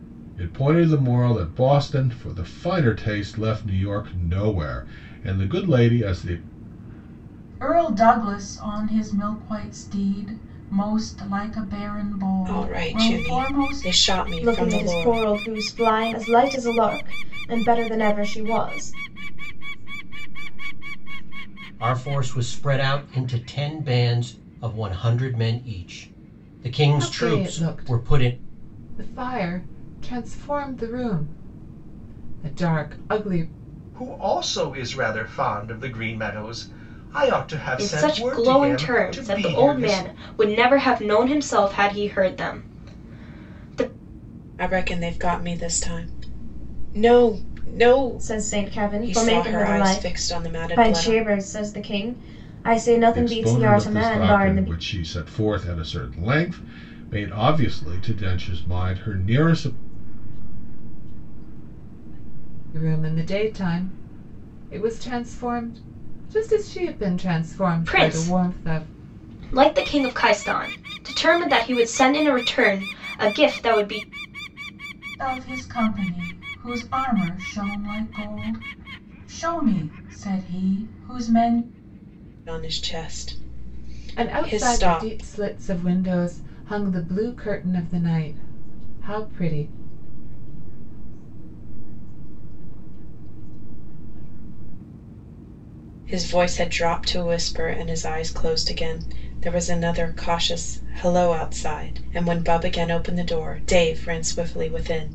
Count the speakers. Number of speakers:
nine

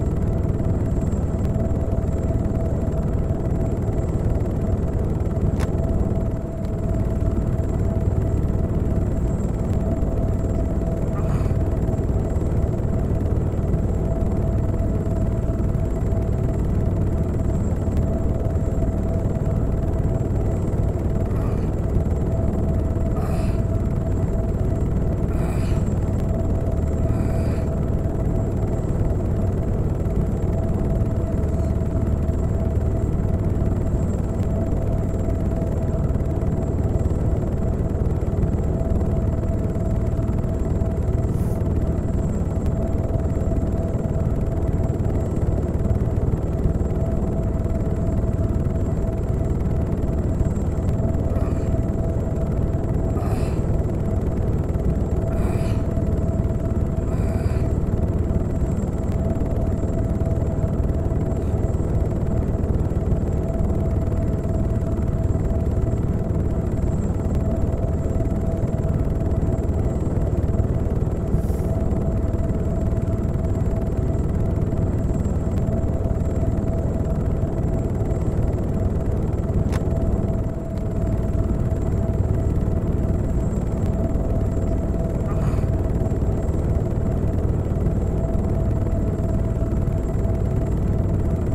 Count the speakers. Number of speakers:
zero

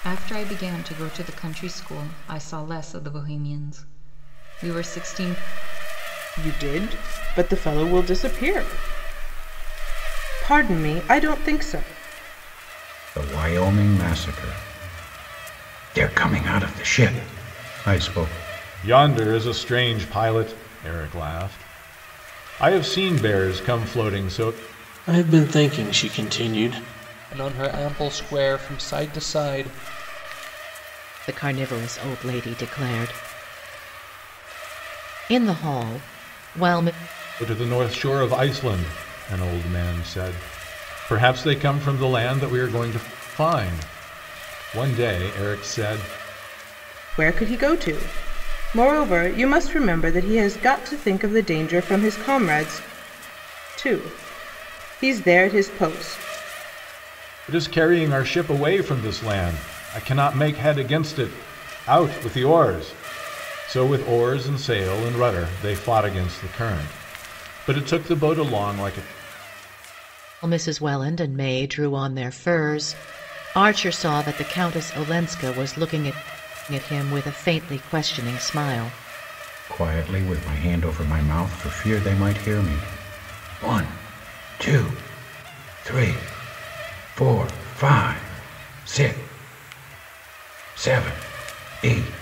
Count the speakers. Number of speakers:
seven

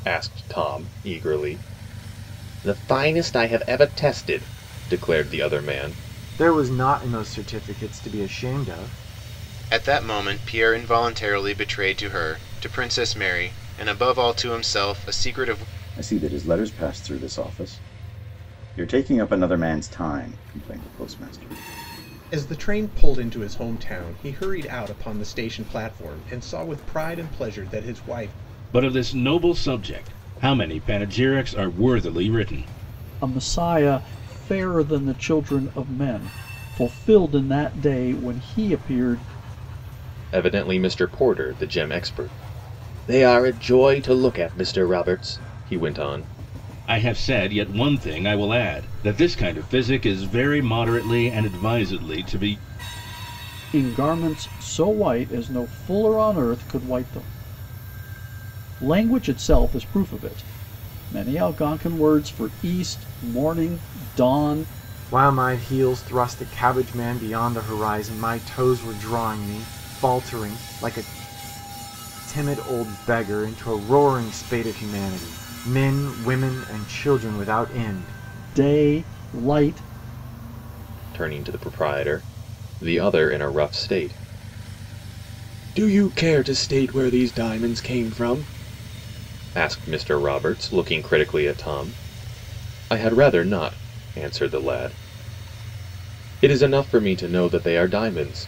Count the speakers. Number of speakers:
seven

